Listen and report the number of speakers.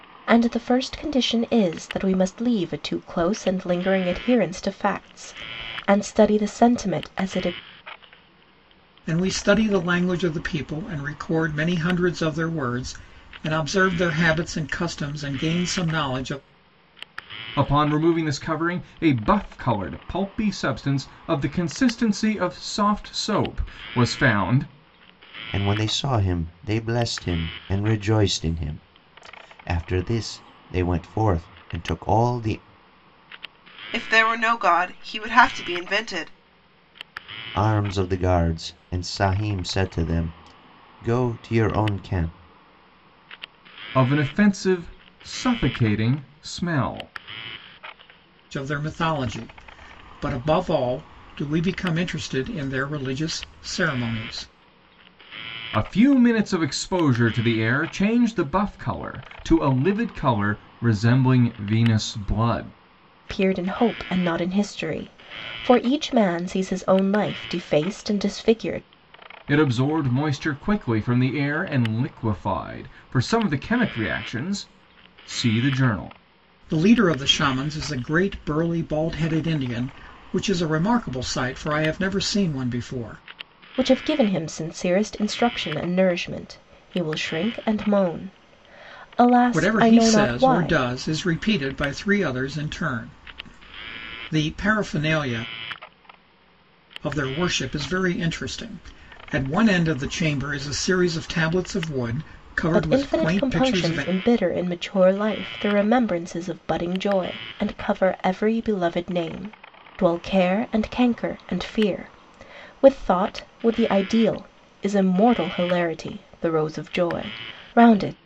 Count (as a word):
five